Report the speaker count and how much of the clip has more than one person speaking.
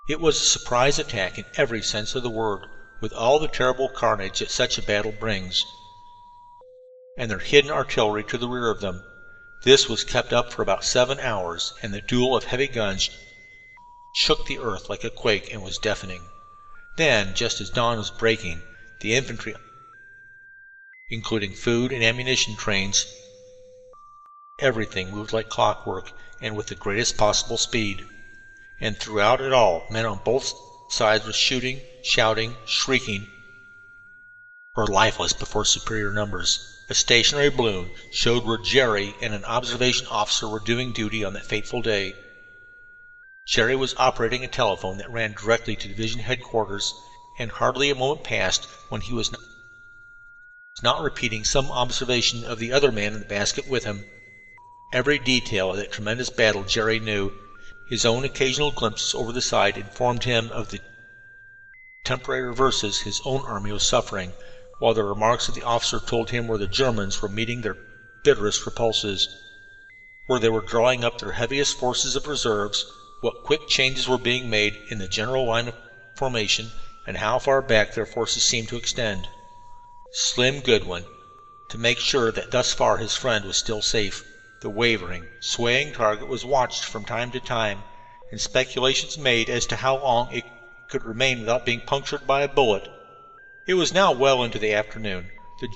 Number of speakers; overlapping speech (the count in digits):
1, no overlap